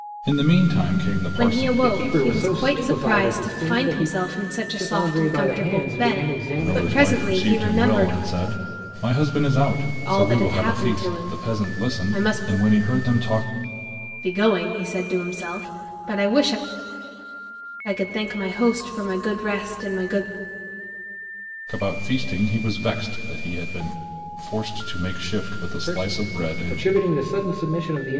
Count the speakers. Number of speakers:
three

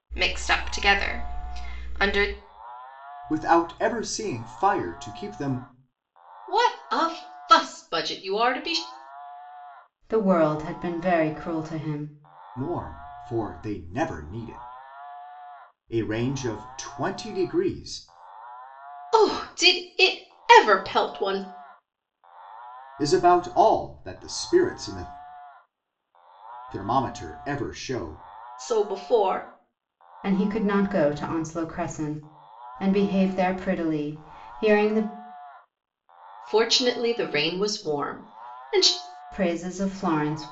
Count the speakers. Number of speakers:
four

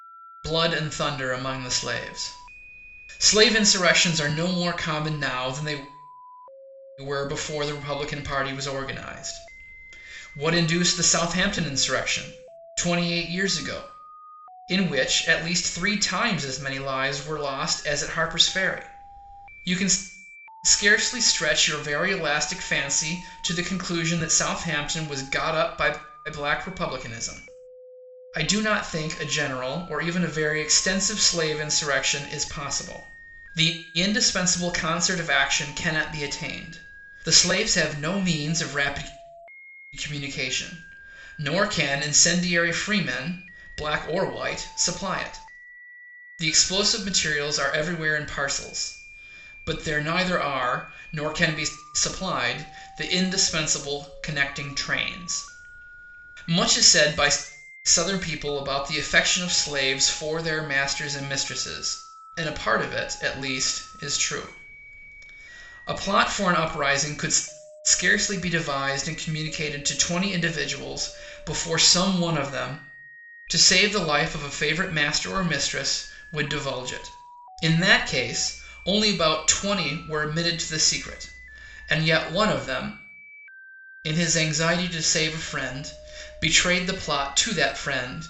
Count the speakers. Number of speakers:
one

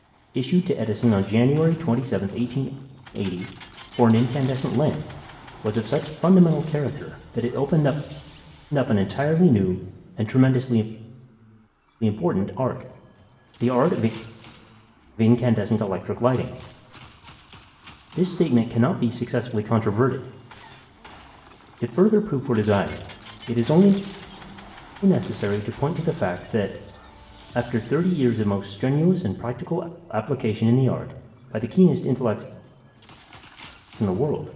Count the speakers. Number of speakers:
one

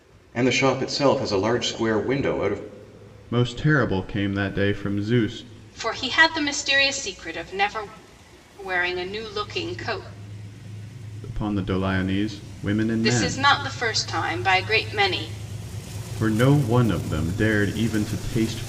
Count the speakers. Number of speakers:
three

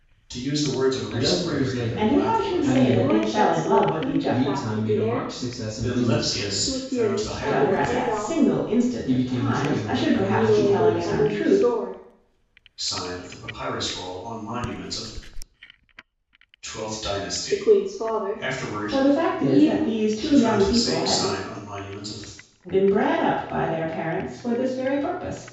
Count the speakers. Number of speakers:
four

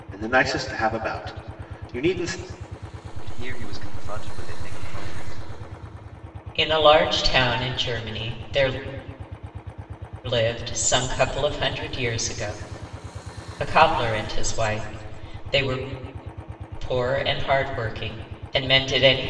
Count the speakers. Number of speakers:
three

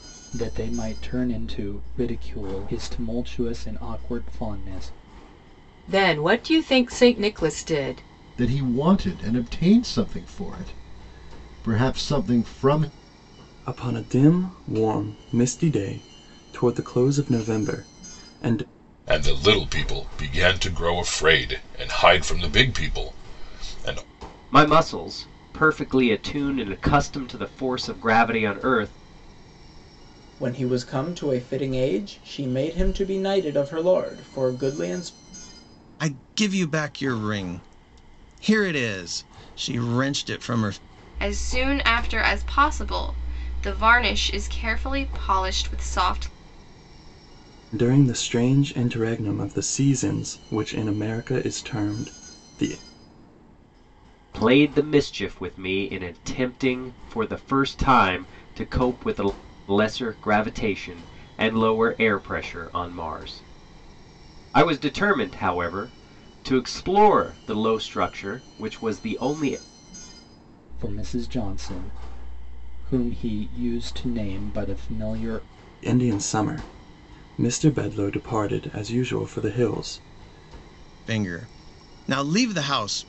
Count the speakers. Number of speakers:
nine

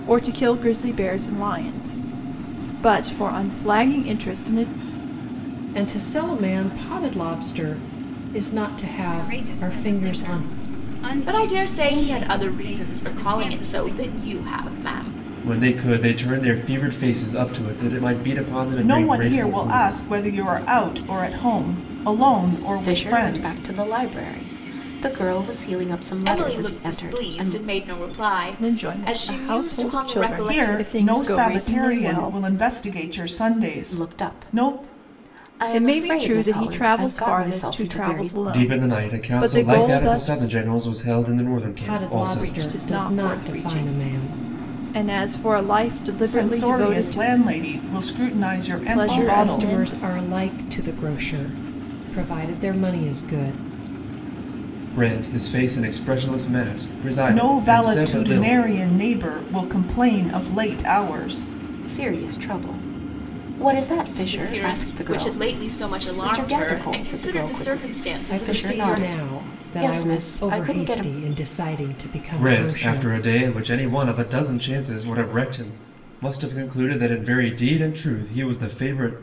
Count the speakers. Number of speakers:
seven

